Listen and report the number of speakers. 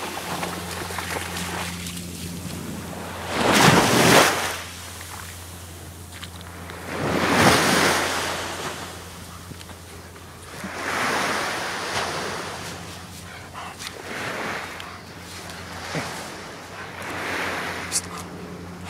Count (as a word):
zero